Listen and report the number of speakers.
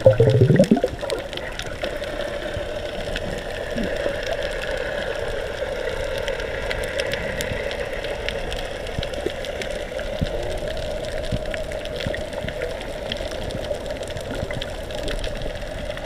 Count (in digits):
0